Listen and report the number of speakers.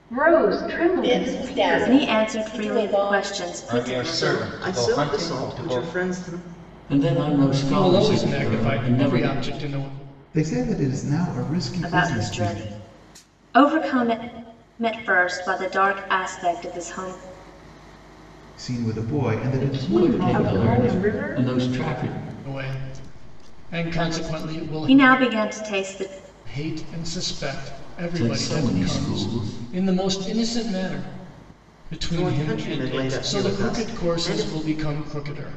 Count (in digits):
8